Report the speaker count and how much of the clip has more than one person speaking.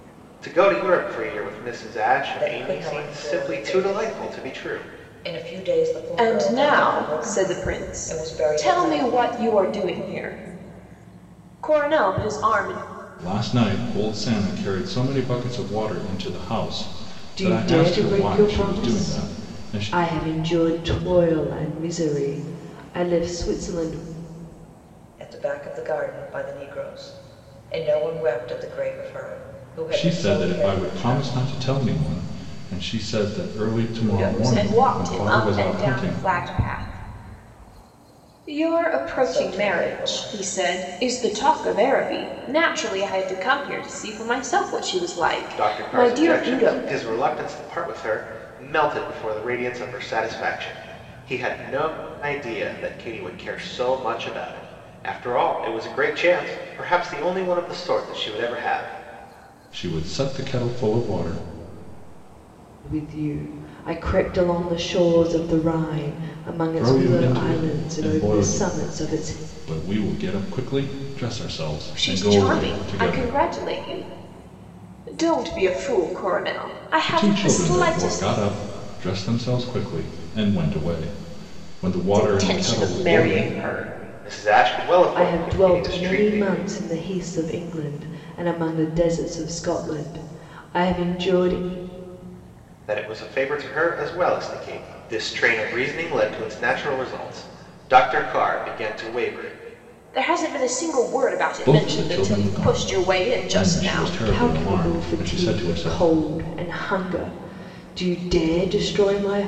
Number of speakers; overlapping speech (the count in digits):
5, about 25%